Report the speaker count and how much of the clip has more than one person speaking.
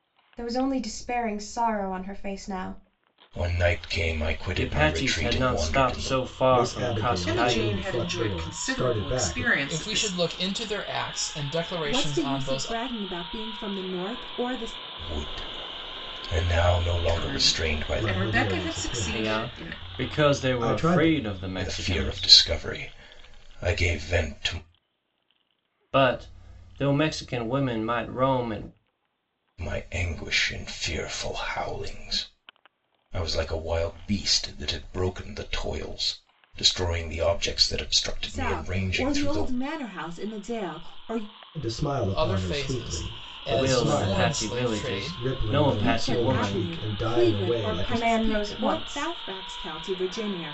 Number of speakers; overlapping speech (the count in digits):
7, about 38%